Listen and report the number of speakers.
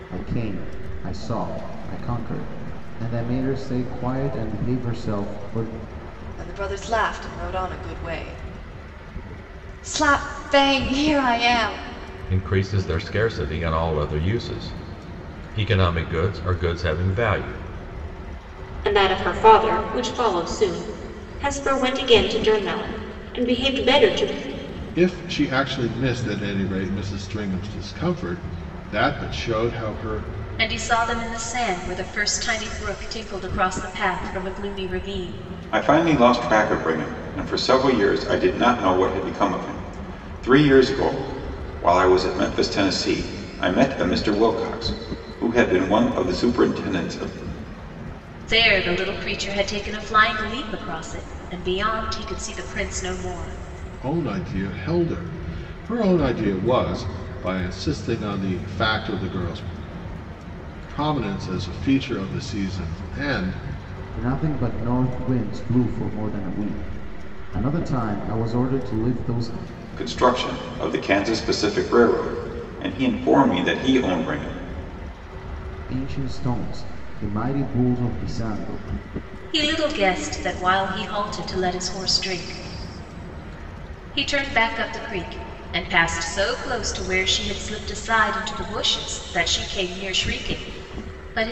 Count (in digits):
7